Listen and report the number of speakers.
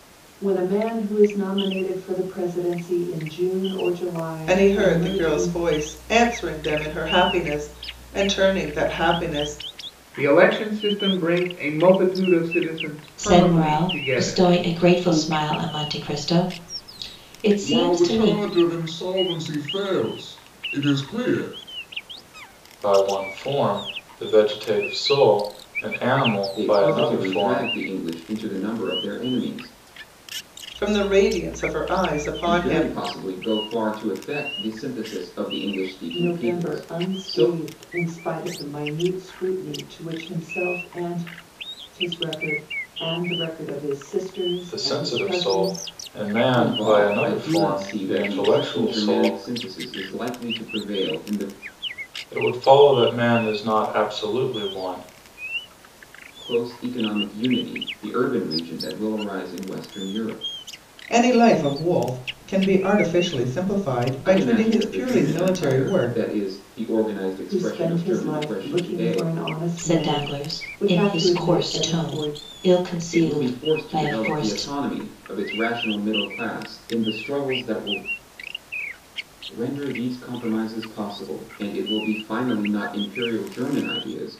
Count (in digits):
7